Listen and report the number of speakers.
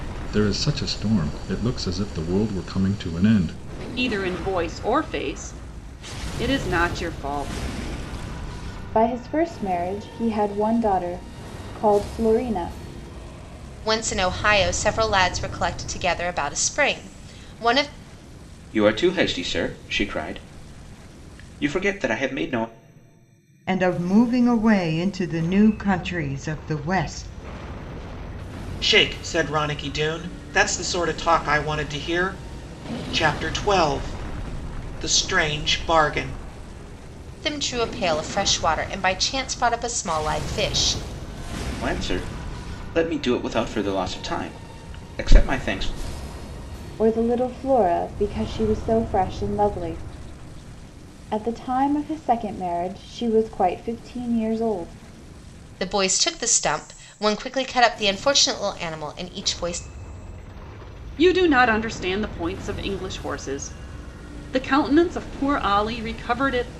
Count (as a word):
seven